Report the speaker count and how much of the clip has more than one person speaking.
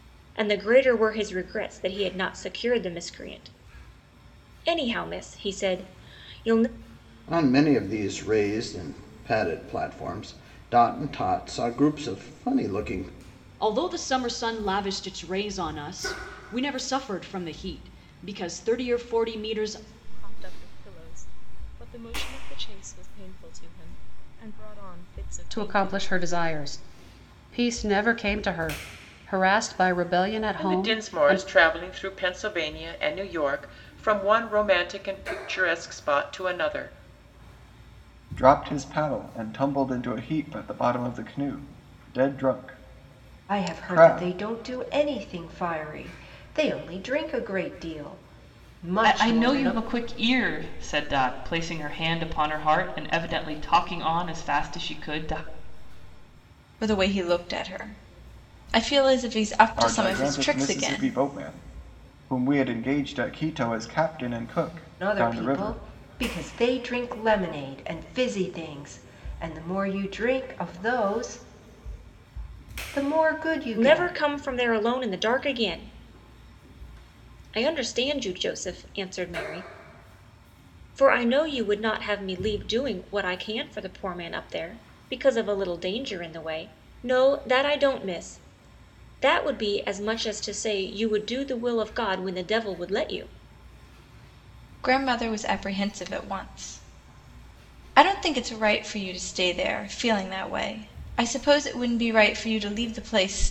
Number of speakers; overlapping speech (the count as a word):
ten, about 6%